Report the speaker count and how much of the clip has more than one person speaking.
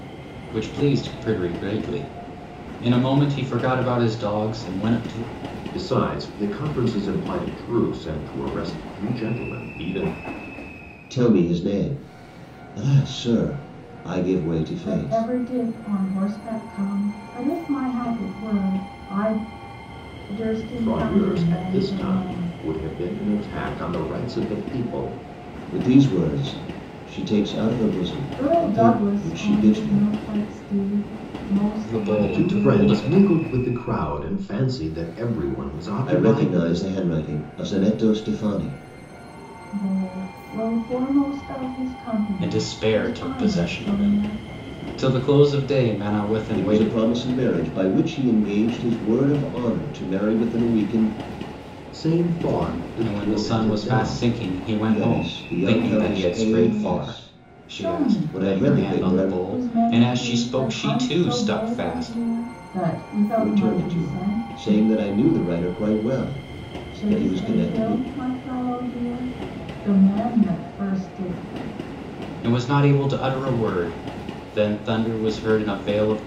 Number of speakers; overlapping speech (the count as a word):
four, about 27%